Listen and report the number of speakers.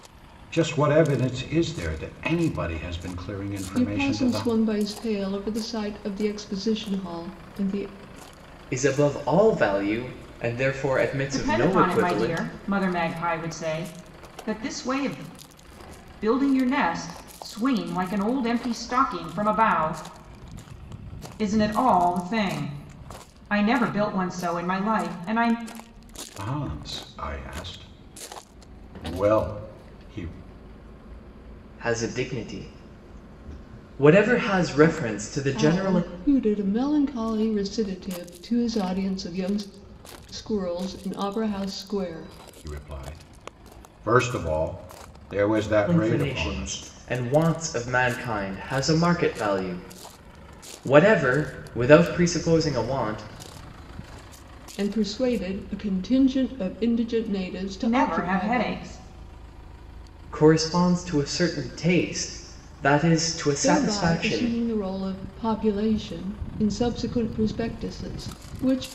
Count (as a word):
four